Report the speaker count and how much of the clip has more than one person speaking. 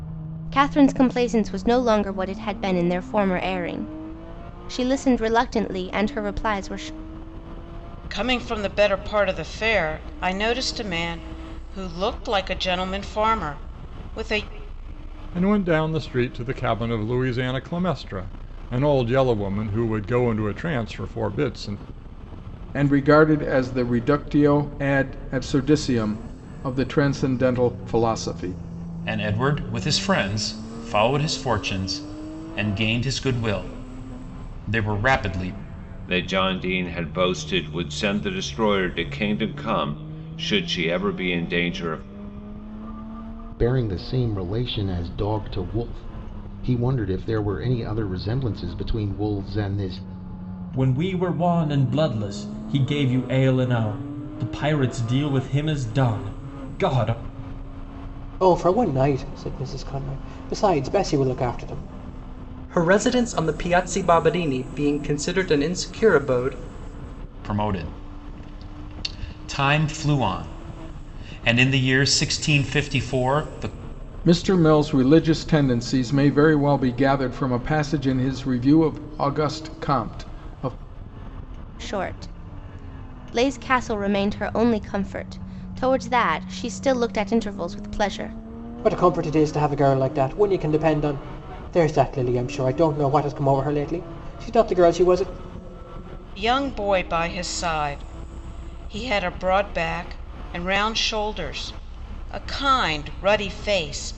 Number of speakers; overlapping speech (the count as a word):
ten, no overlap